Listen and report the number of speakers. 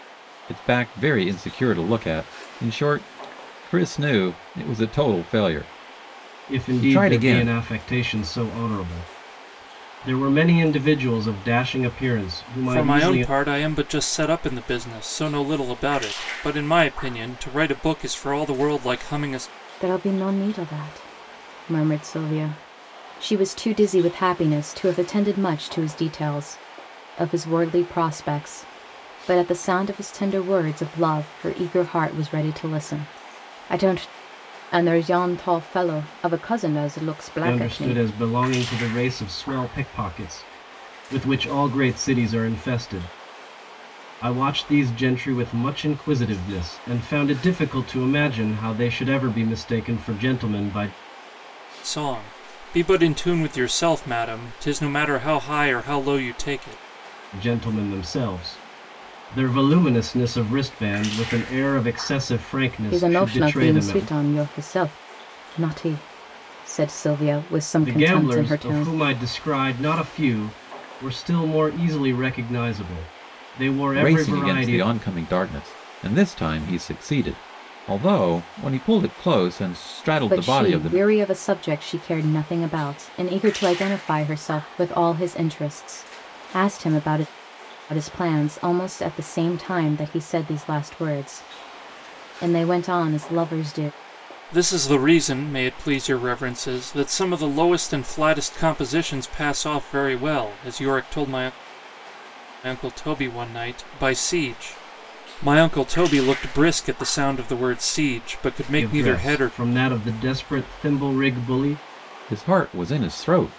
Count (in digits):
4